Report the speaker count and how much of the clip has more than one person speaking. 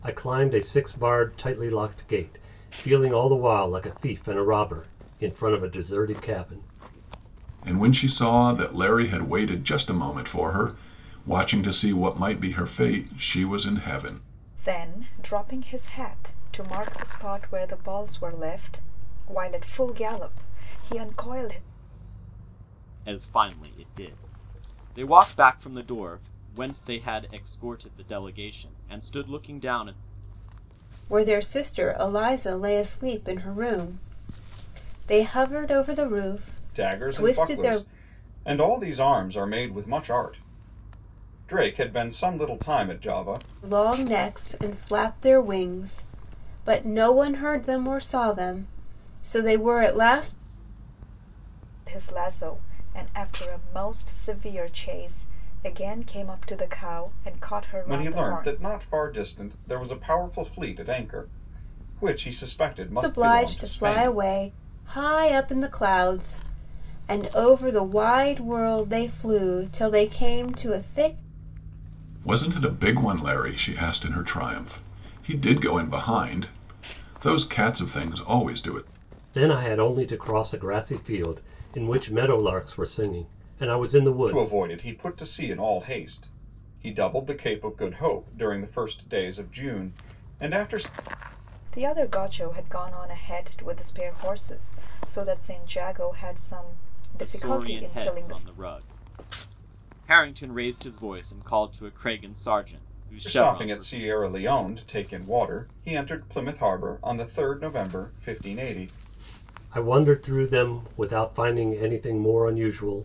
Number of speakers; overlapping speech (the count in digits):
6, about 5%